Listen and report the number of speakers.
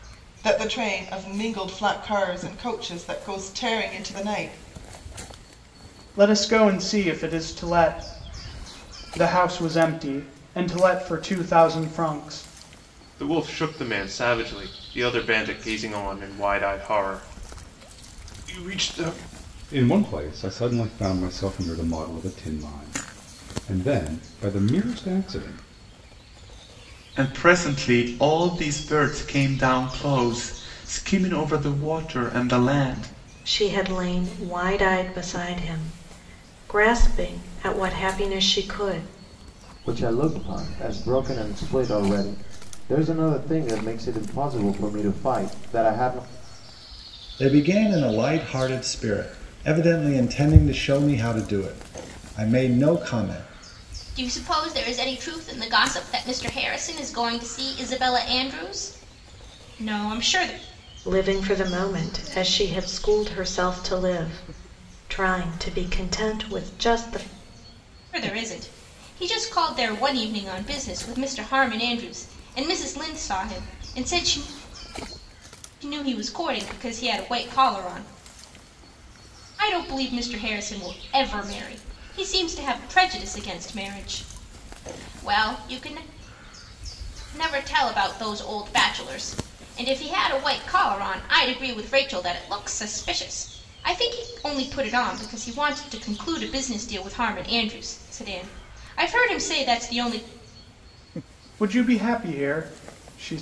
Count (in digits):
9